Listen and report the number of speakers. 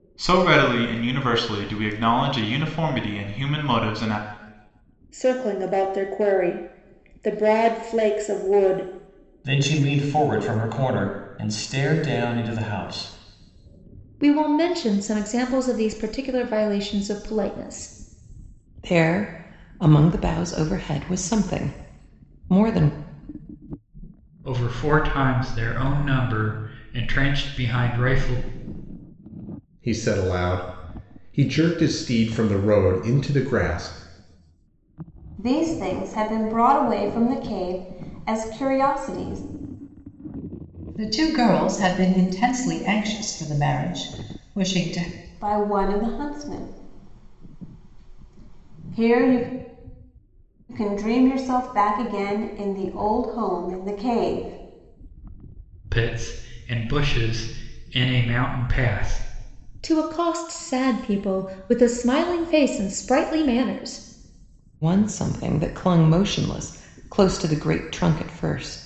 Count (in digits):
9